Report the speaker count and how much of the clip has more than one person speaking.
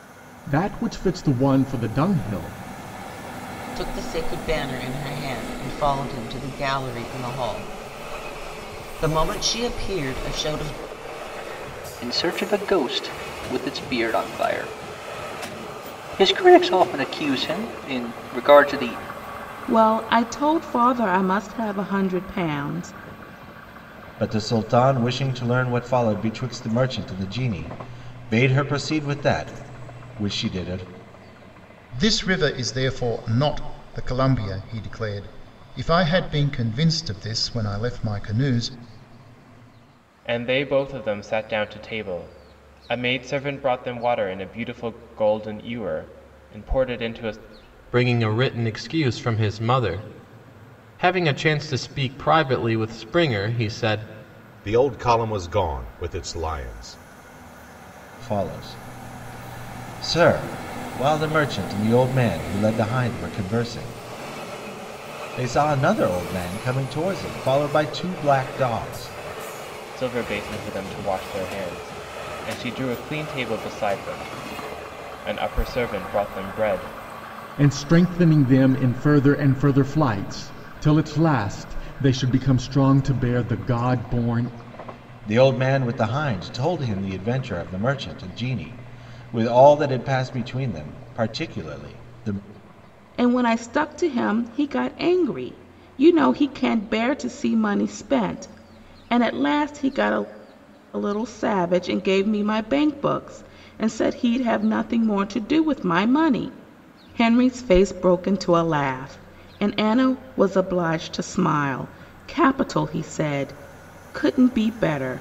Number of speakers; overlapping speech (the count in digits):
9, no overlap